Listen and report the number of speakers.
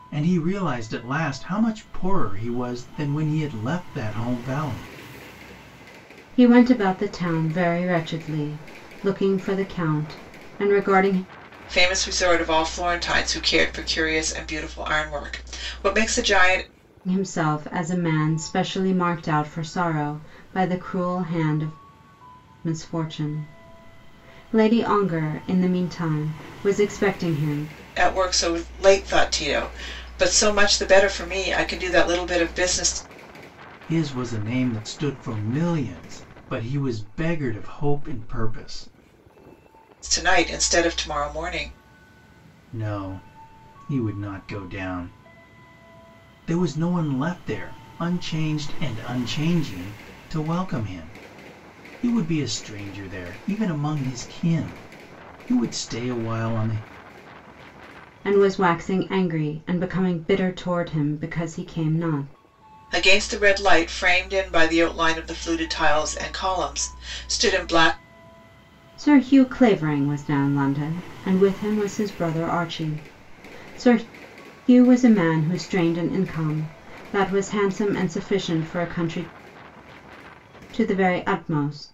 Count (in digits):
3